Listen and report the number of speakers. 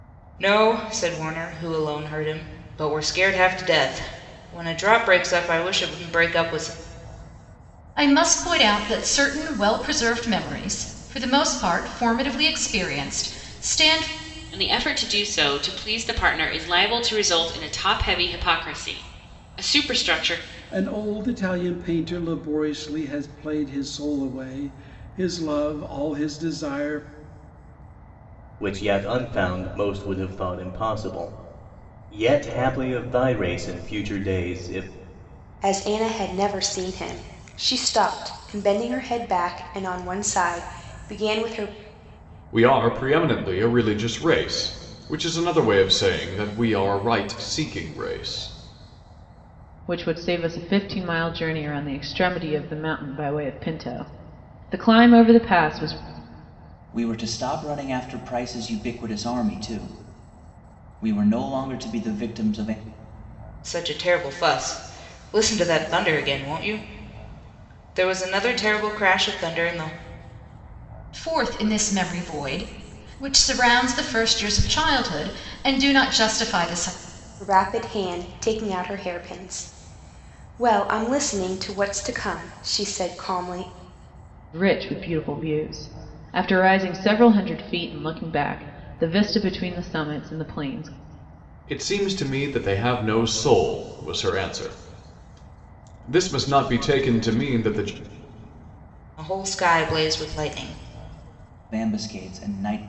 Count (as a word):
nine